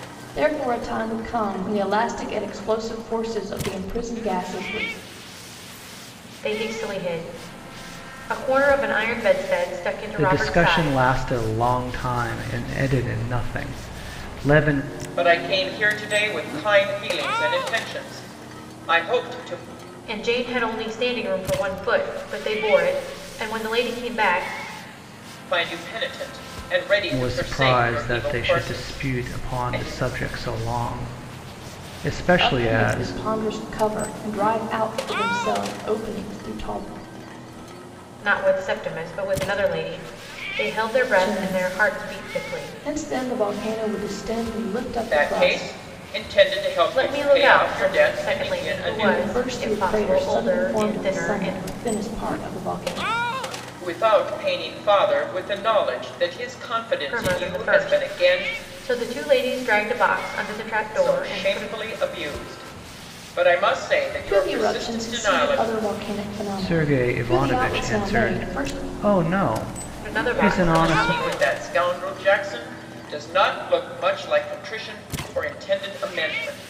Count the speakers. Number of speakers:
four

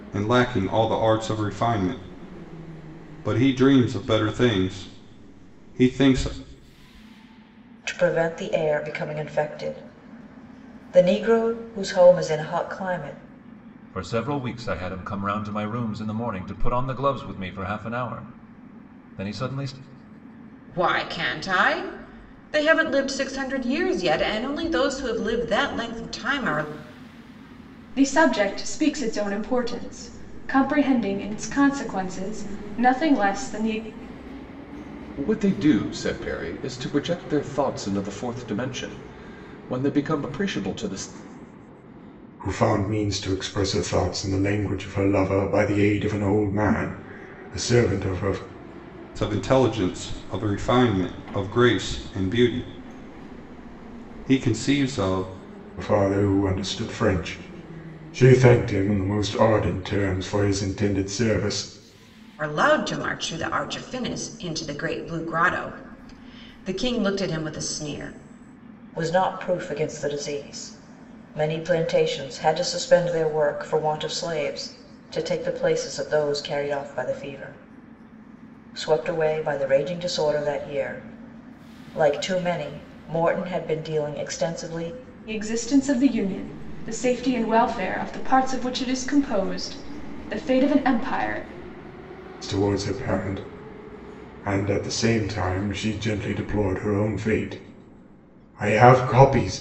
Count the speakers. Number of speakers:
seven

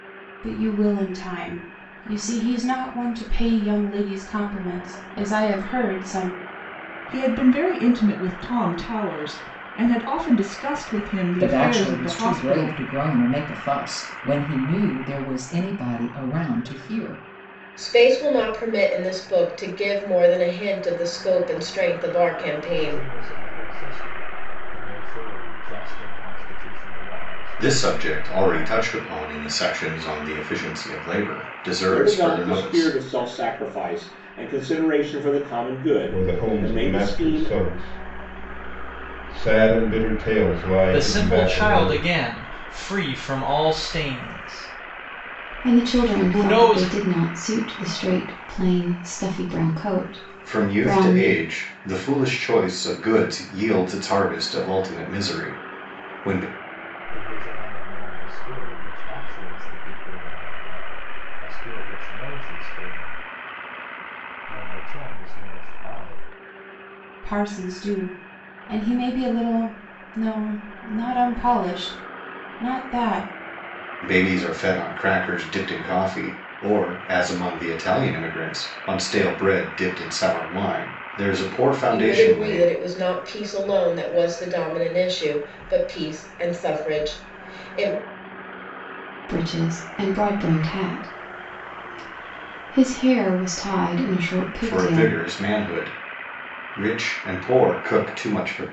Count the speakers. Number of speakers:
ten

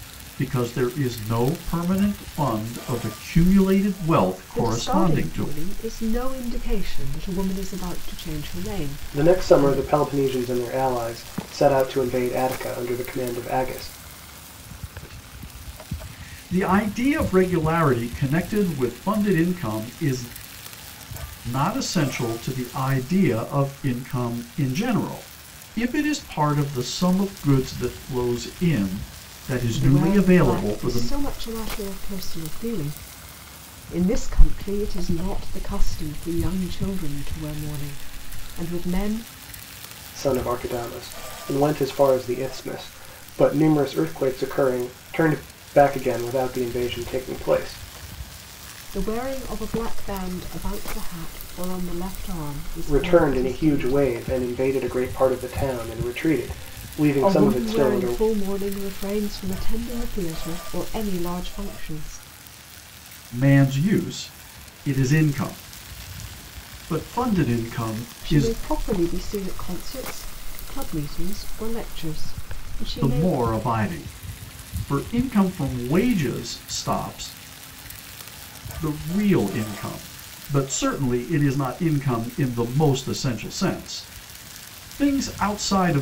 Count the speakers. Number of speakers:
three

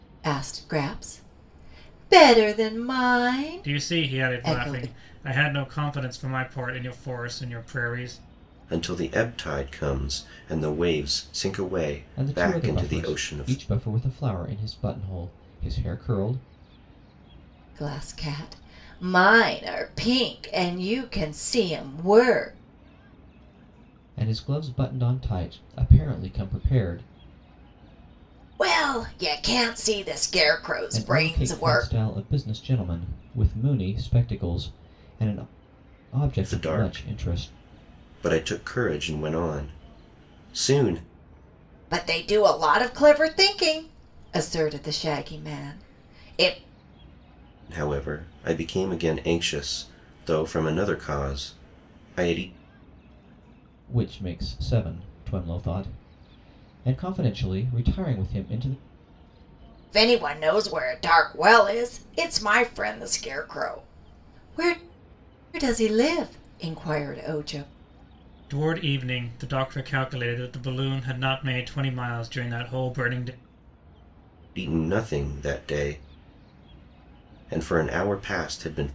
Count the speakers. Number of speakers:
four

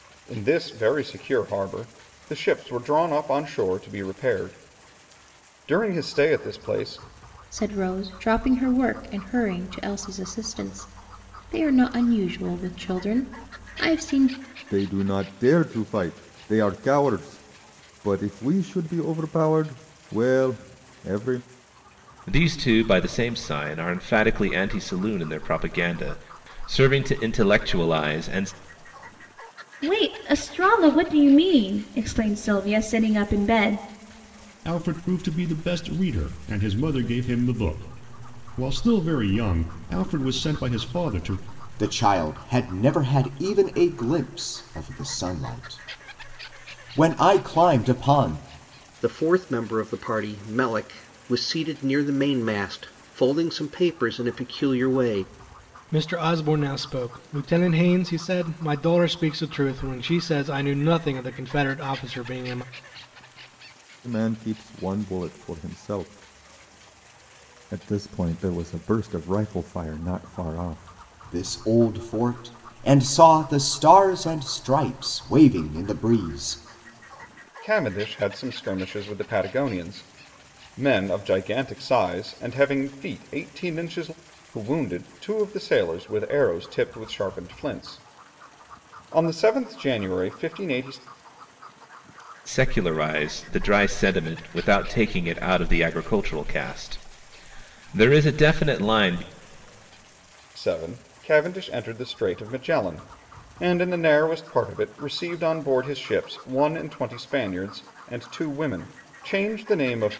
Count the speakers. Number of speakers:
nine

